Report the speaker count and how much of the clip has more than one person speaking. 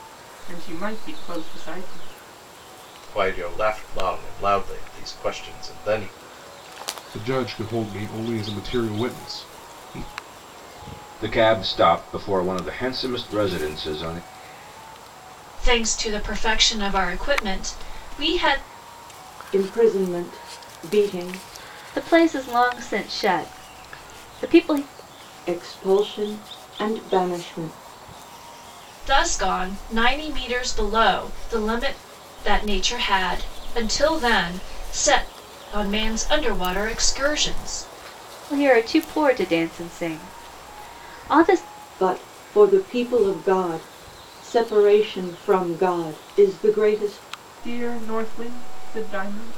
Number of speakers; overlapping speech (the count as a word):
seven, no overlap